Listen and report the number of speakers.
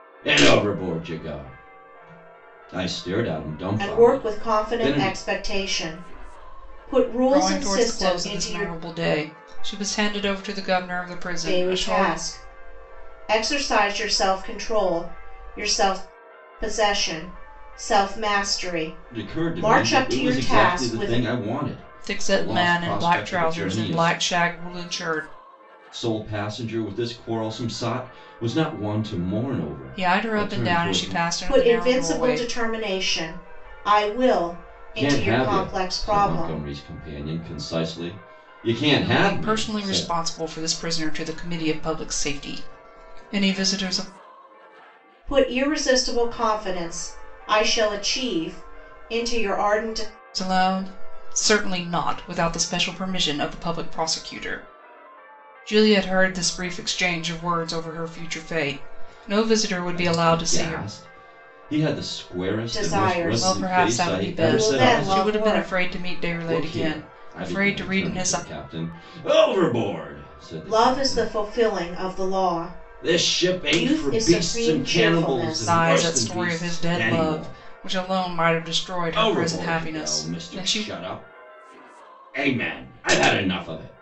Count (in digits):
3